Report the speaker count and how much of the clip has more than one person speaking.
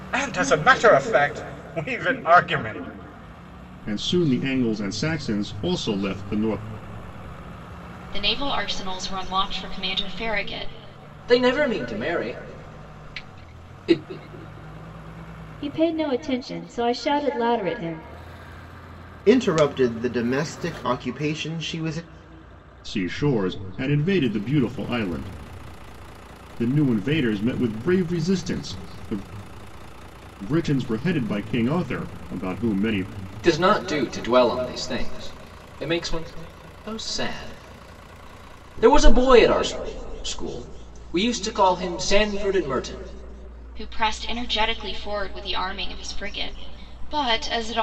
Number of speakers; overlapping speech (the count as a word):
six, no overlap